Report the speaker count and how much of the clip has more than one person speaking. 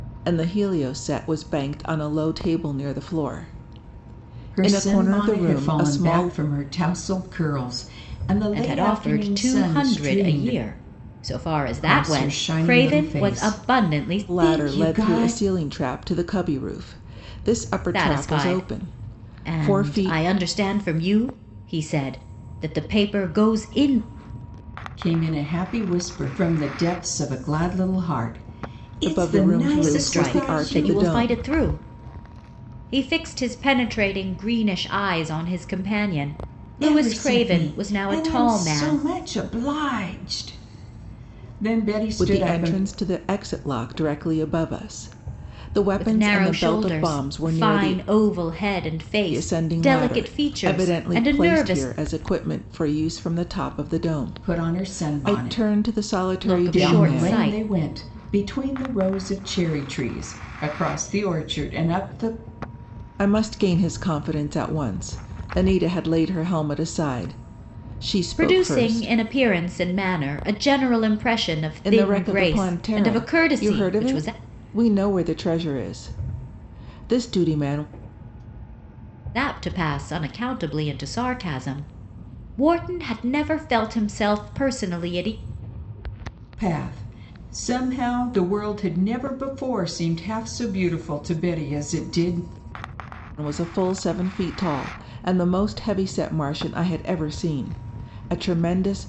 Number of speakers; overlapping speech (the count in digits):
3, about 26%